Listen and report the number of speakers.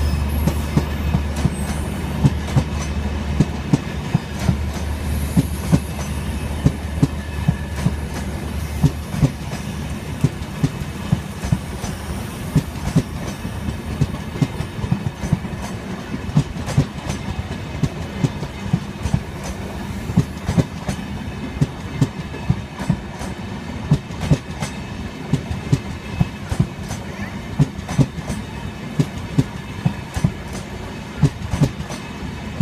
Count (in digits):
0